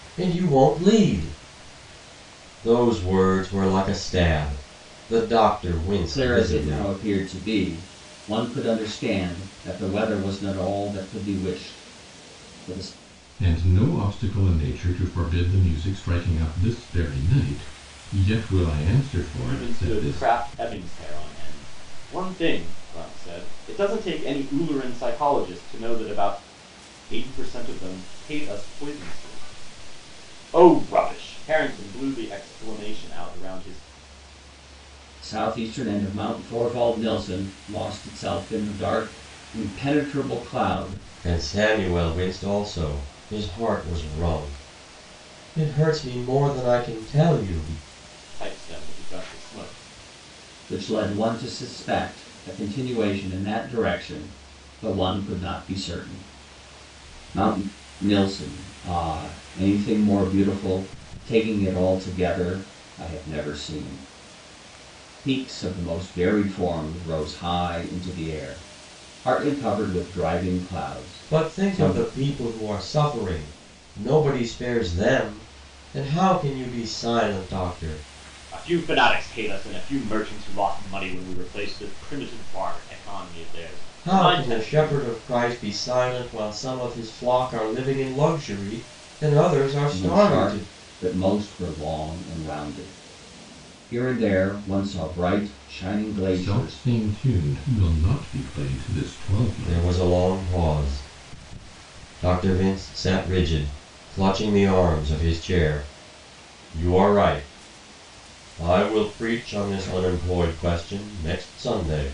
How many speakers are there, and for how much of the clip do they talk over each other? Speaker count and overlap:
four, about 5%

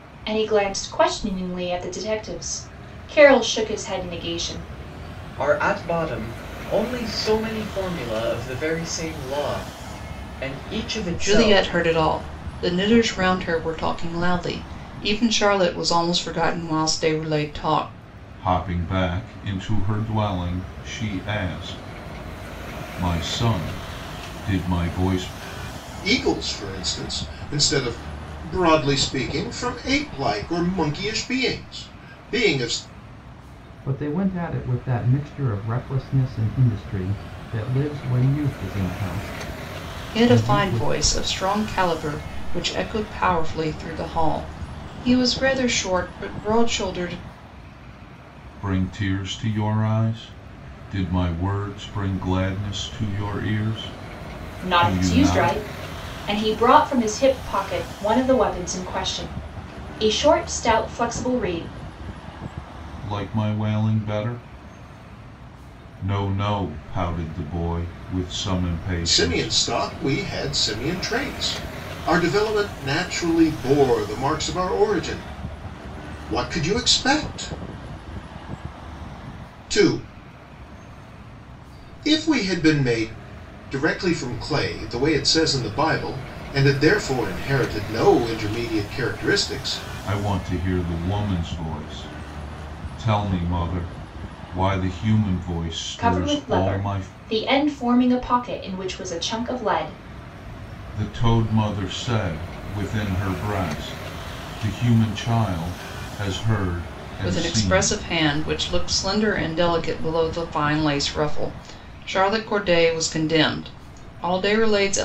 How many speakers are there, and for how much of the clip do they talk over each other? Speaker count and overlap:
six, about 4%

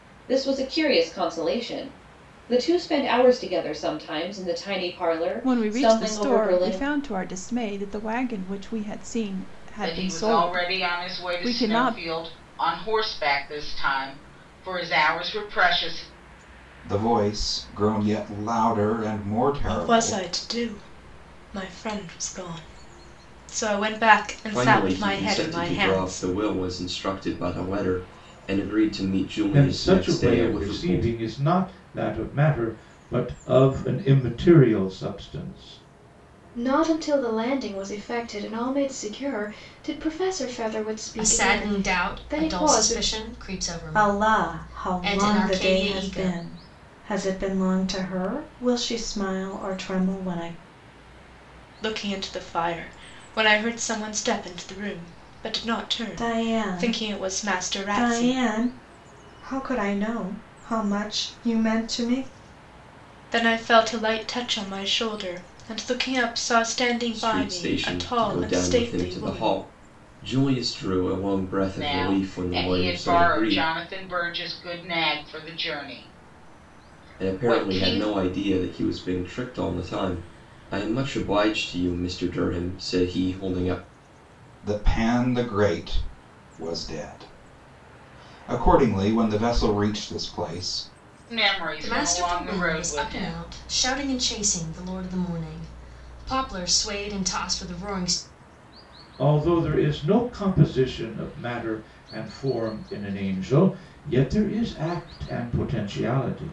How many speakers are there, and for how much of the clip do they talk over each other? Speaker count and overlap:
ten, about 20%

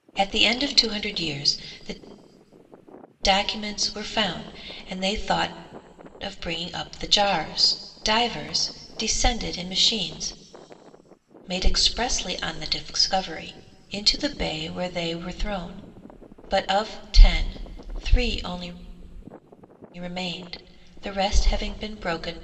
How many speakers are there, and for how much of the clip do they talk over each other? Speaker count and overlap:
one, no overlap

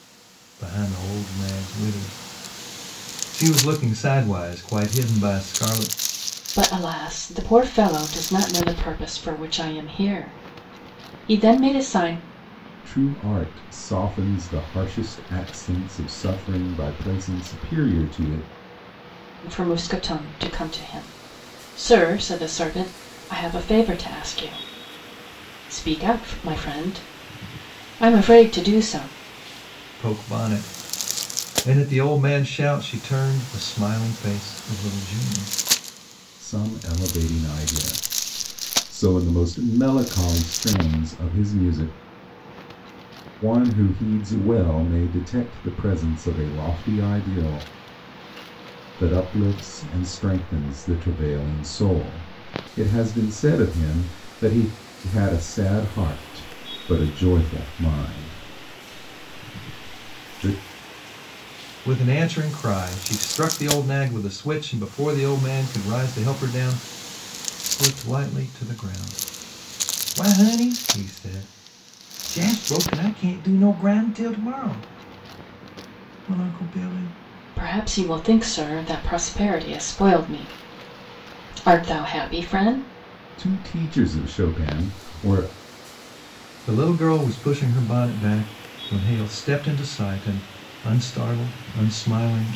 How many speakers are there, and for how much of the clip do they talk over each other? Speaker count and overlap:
three, no overlap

